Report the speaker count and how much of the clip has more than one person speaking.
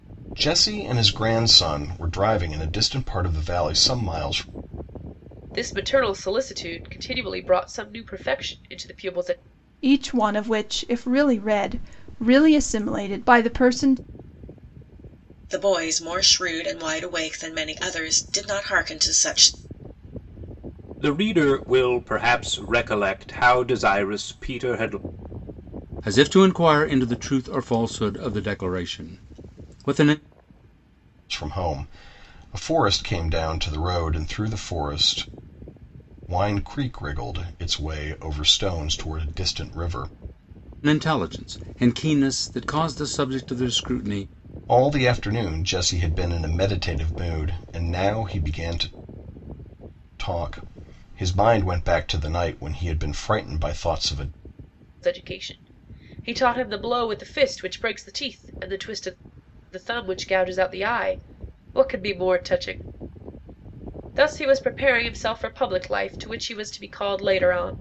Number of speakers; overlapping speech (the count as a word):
six, no overlap